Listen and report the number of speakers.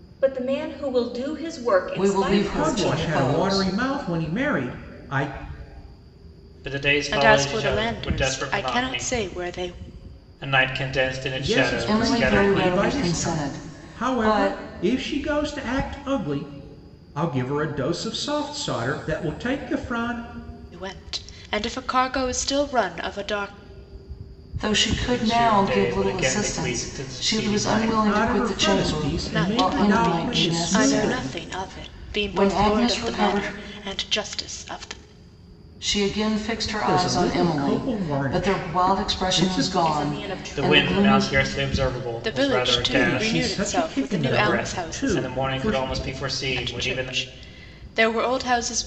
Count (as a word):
five